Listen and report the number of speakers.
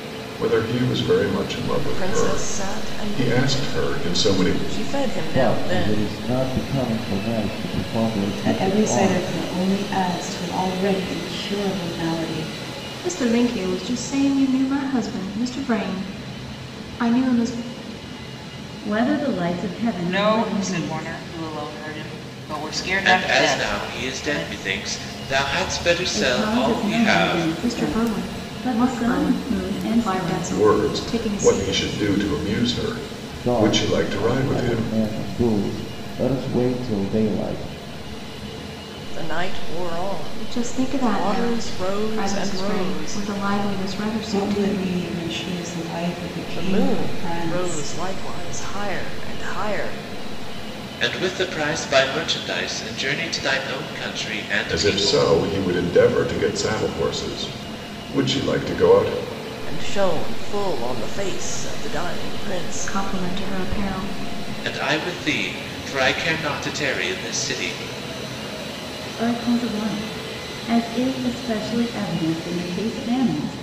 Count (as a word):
eight